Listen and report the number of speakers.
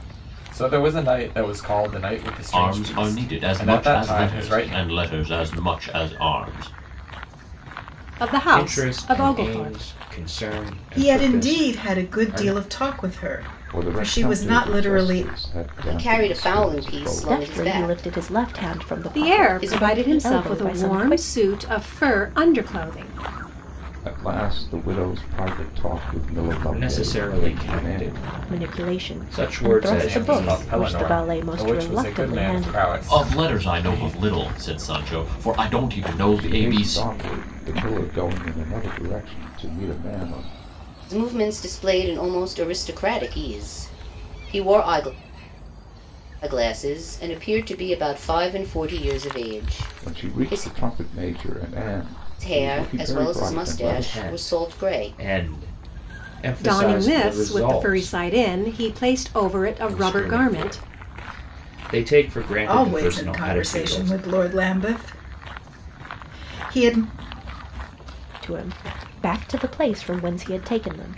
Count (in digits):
8